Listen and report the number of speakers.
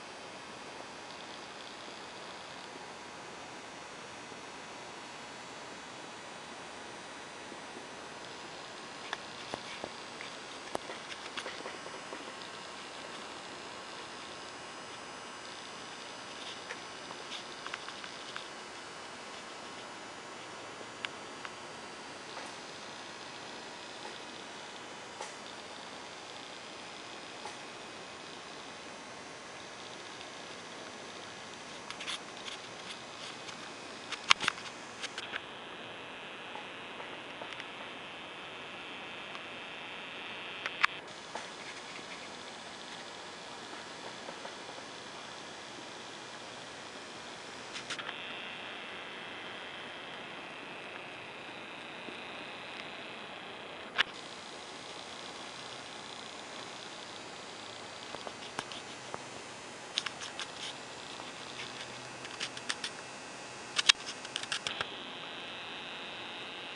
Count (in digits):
0